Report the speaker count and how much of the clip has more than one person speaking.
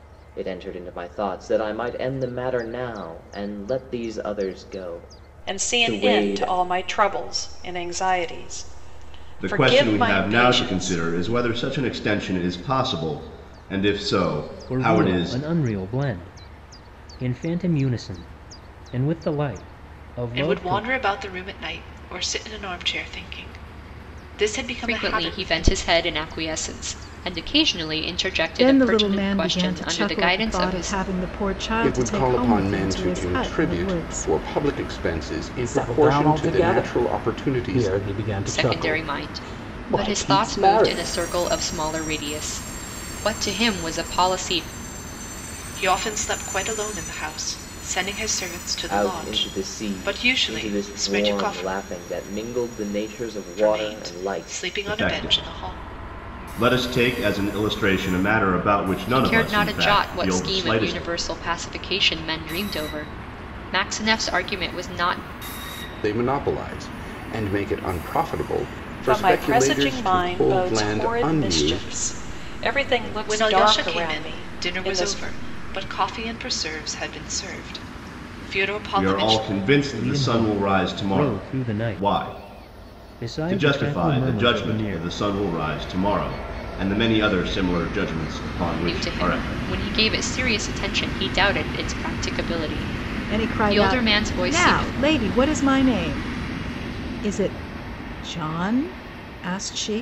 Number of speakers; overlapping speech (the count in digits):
9, about 34%